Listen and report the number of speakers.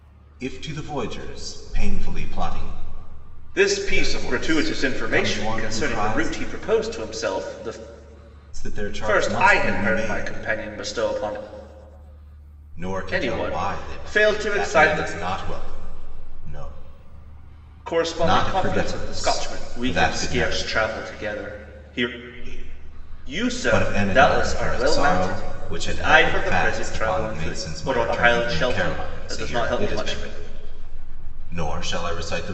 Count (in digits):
2